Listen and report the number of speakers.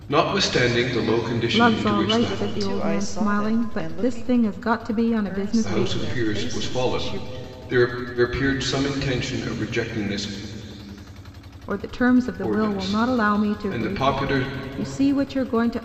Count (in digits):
3